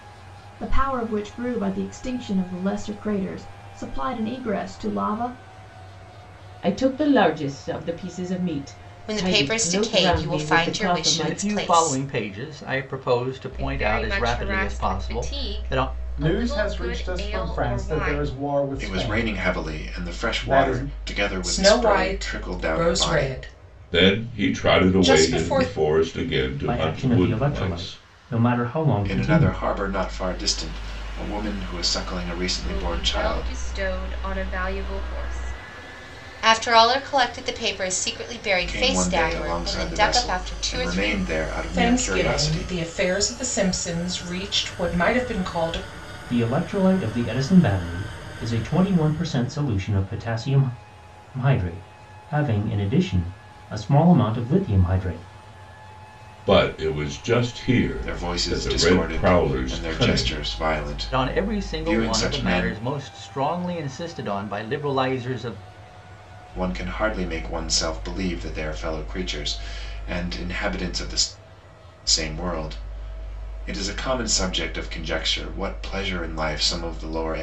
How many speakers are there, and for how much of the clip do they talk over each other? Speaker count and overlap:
10, about 31%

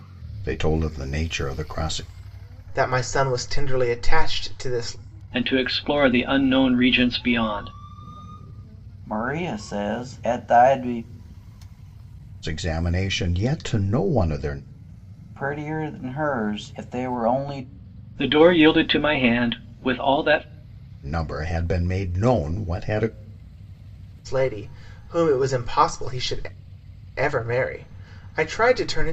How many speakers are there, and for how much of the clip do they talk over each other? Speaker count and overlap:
4, no overlap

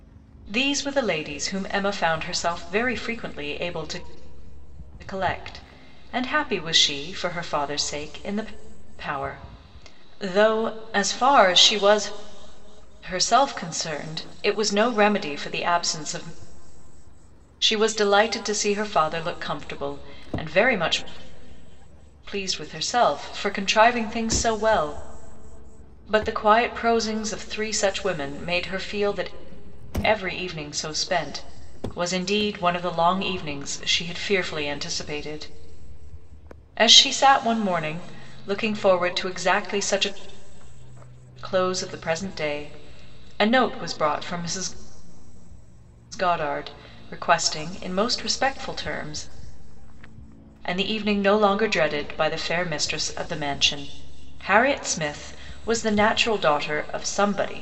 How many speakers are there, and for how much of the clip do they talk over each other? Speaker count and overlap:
1, no overlap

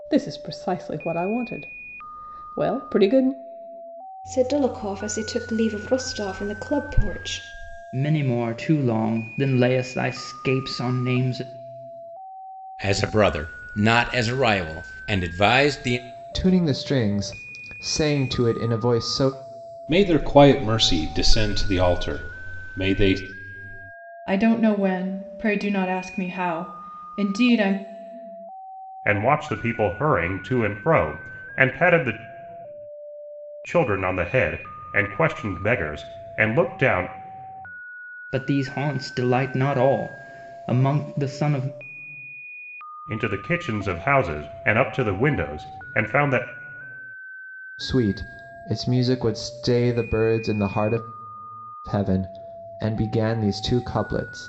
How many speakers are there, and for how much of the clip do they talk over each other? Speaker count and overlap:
8, no overlap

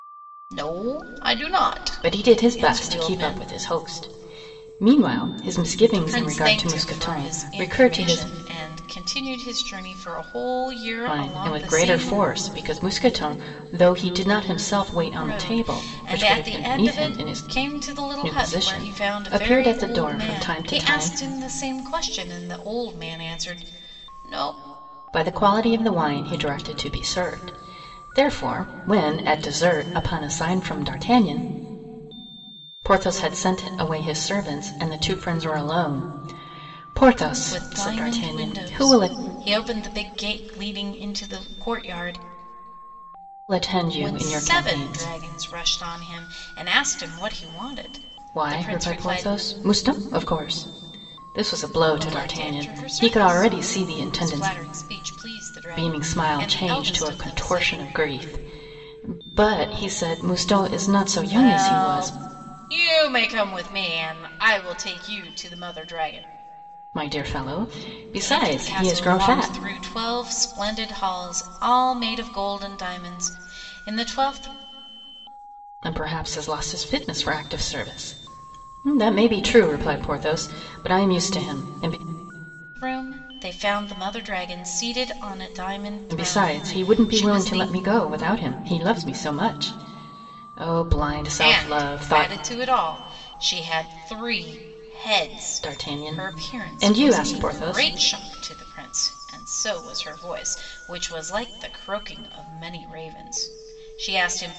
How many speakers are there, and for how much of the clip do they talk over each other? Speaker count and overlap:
2, about 25%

